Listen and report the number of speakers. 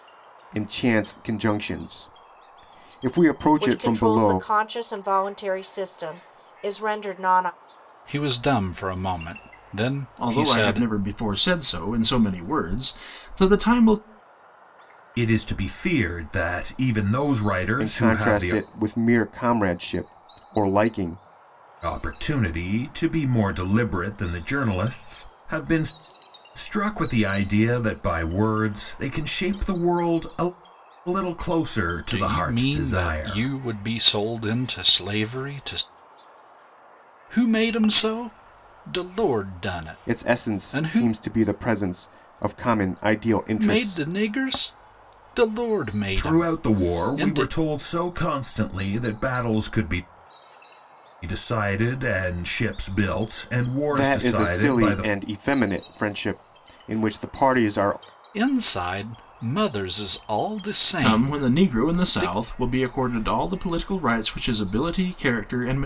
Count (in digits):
5